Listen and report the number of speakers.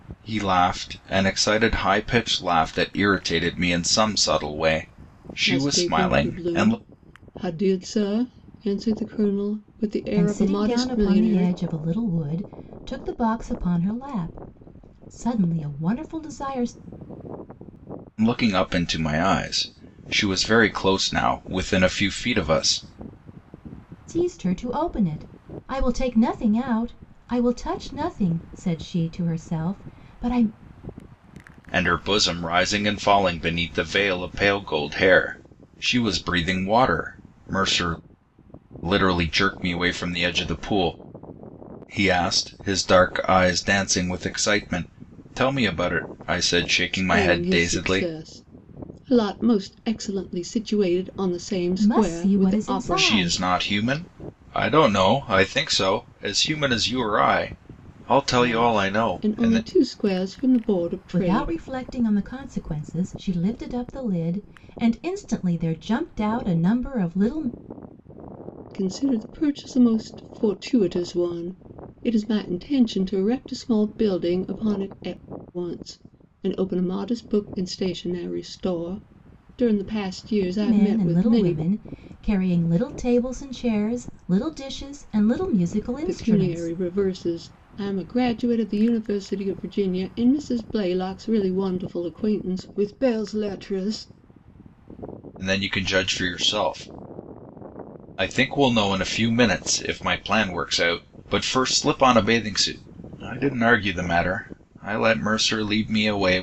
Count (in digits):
3